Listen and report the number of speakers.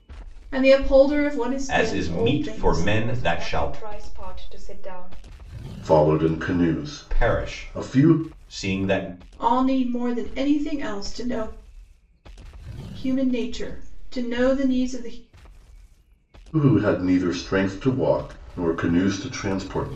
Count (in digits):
4